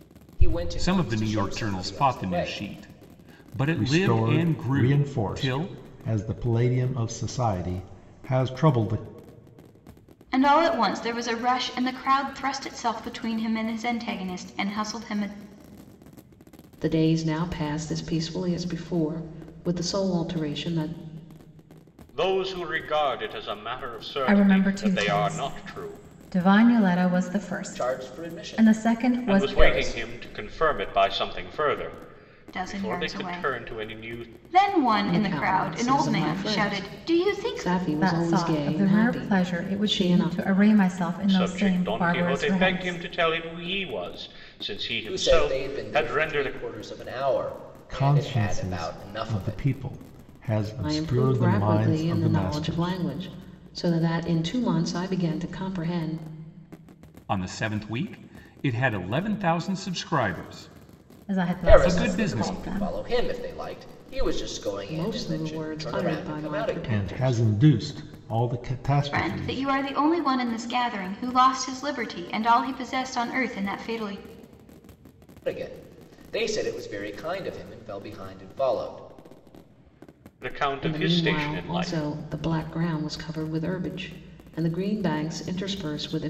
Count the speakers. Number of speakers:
7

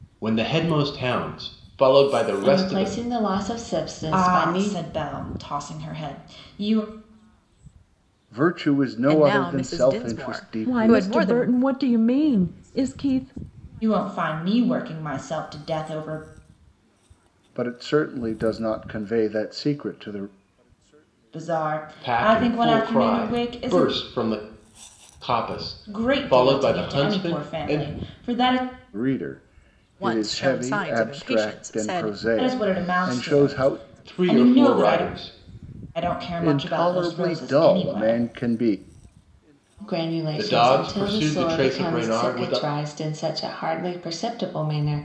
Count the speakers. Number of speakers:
6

